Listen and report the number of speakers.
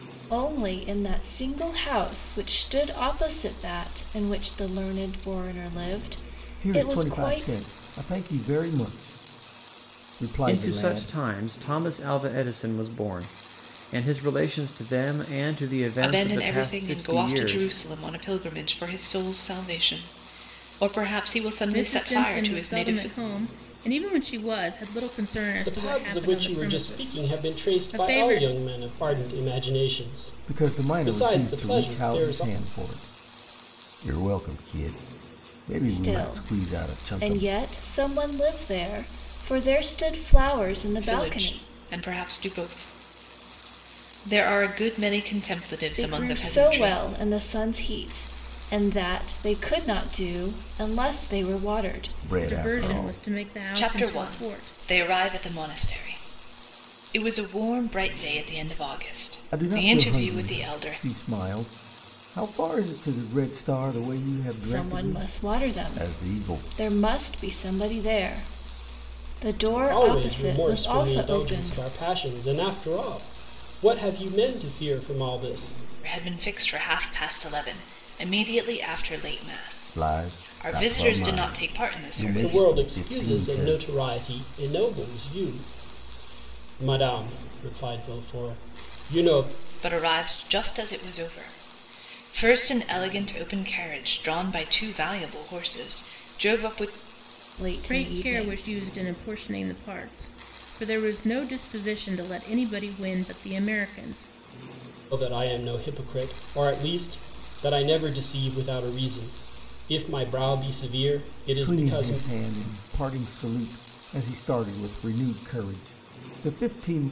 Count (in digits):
6